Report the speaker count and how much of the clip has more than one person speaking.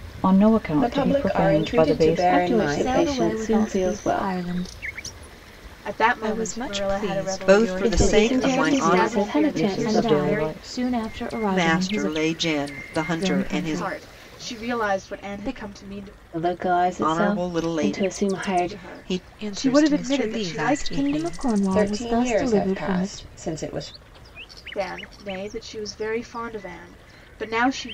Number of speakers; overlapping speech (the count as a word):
seven, about 61%